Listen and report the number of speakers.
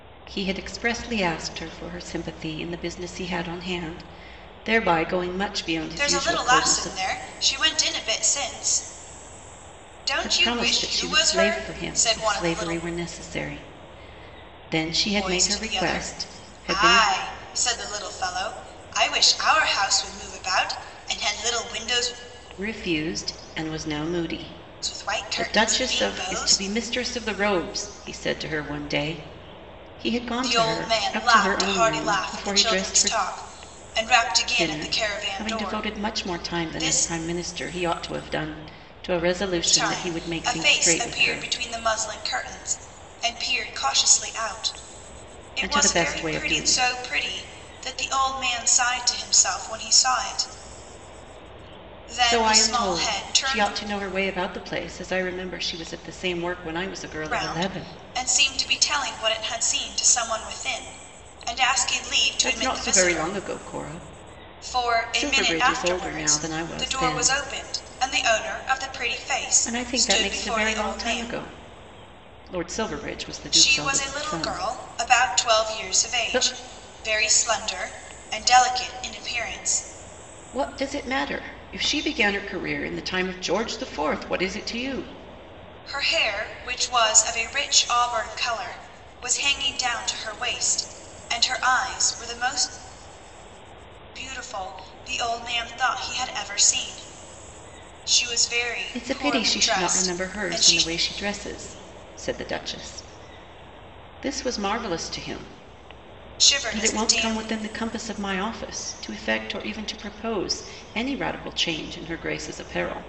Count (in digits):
2